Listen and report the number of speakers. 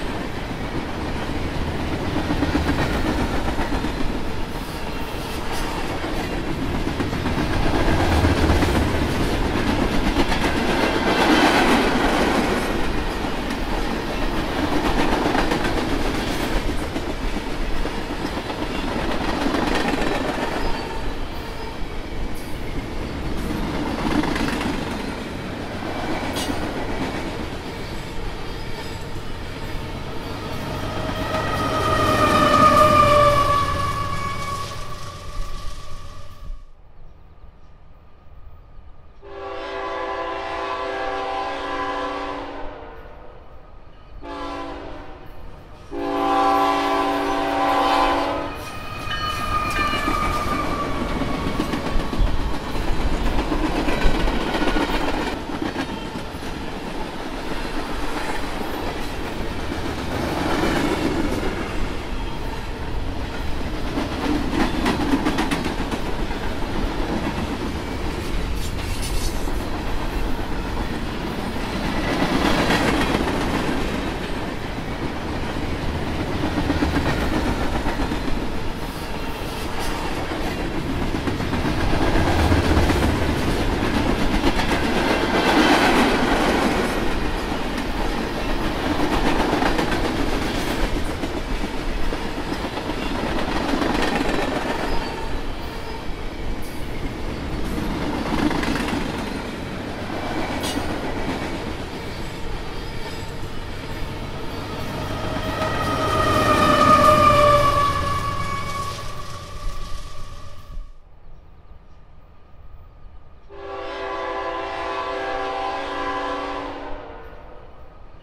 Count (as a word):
zero